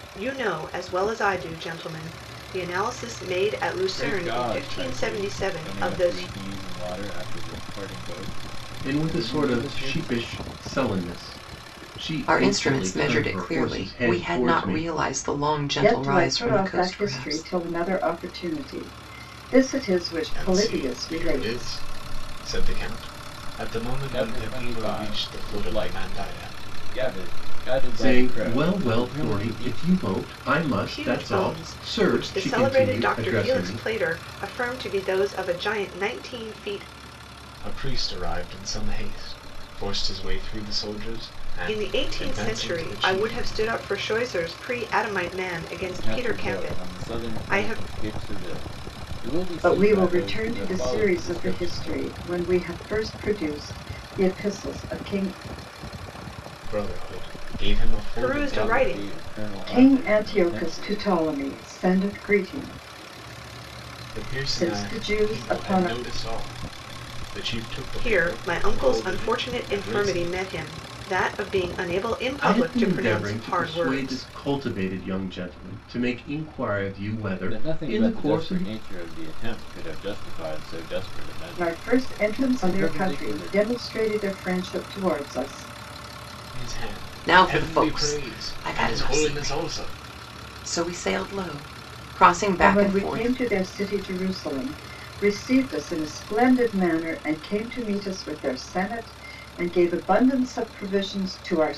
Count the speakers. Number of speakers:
6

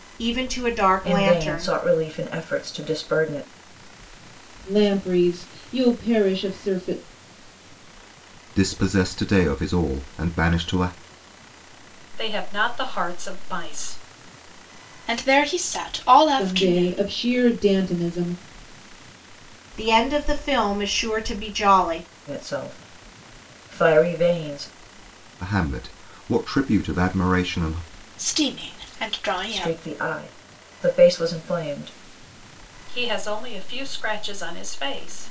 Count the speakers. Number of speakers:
6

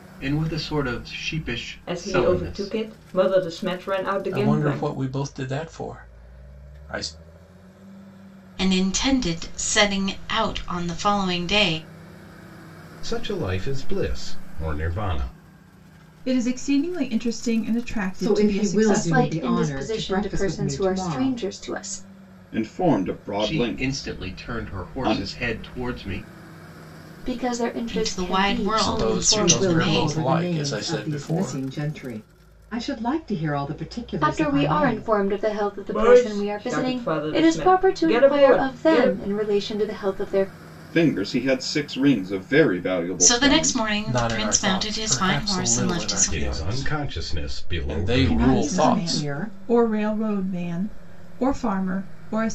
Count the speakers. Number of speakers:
9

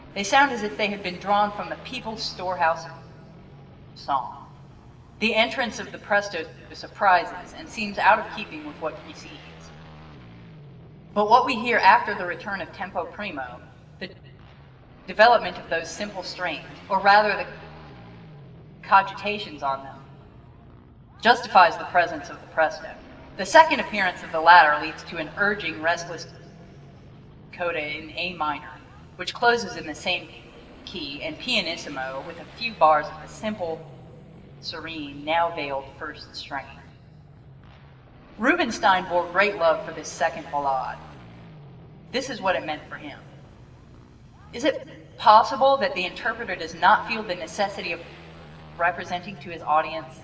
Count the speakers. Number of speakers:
1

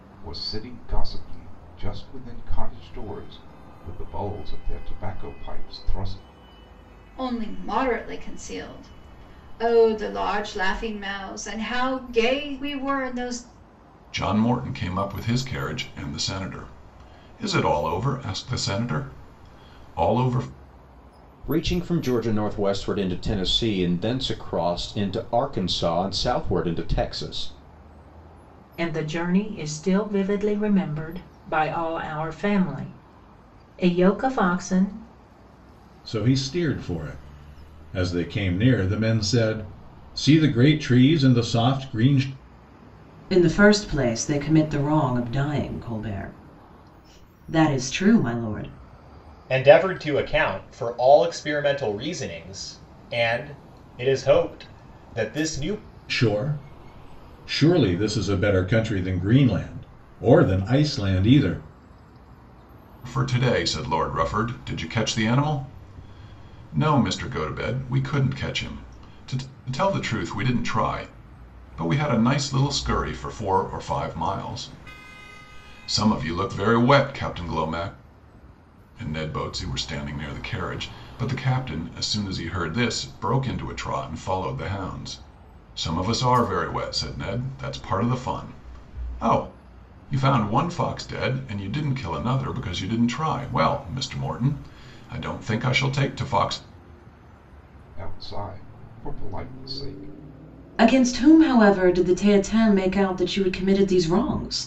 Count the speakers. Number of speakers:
8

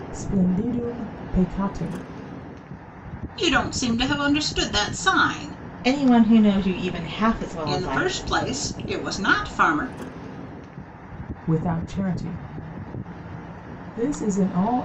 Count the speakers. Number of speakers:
3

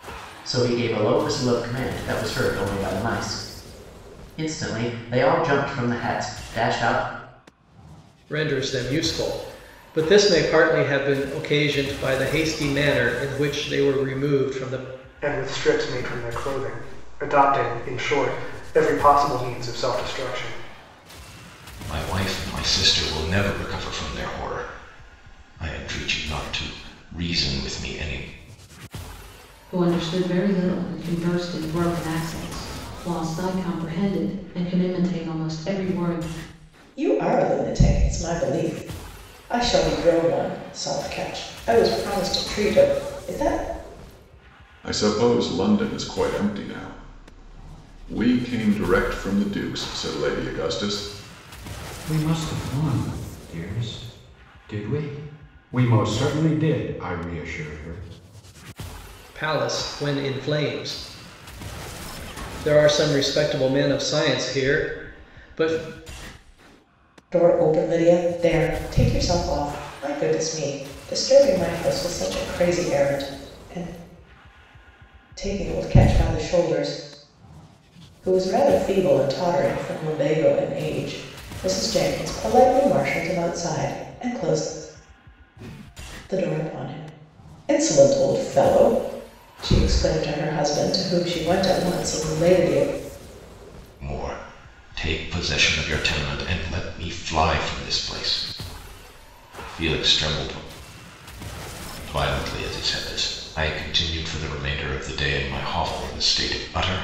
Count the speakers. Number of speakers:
8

